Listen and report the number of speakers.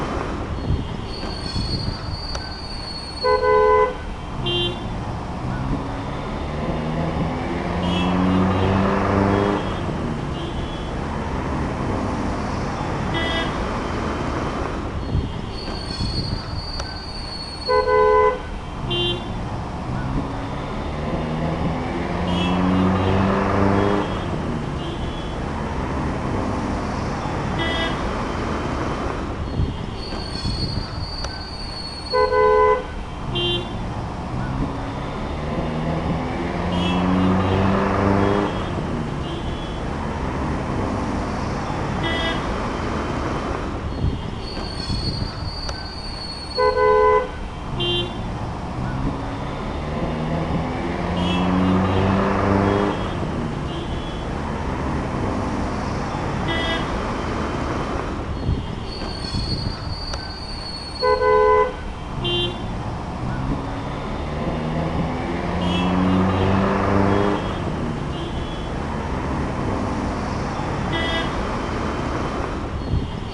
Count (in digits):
0